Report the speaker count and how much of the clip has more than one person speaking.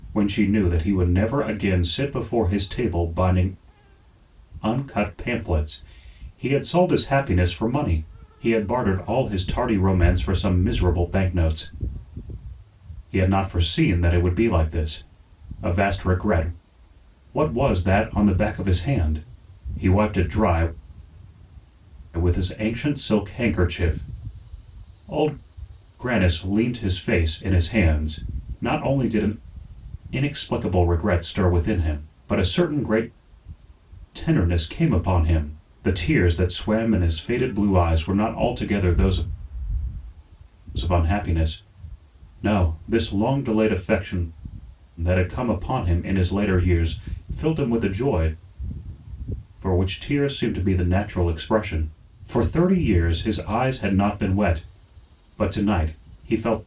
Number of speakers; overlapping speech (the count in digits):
1, no overlap